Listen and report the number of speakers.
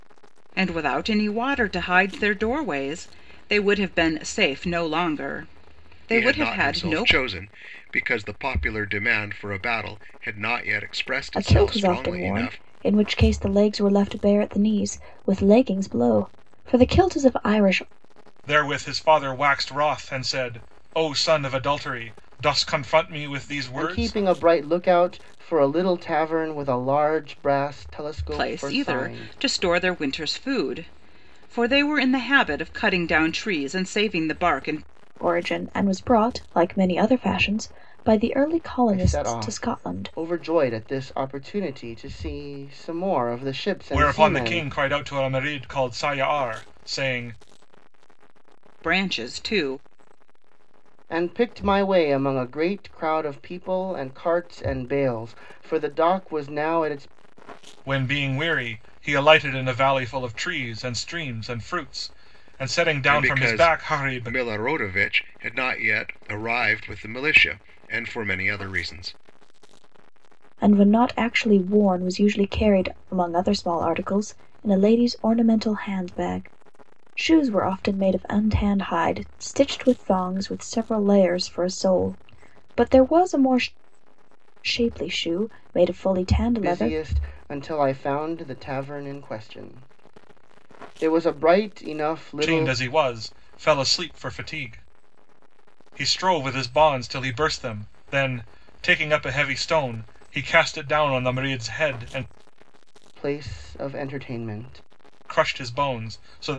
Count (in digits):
5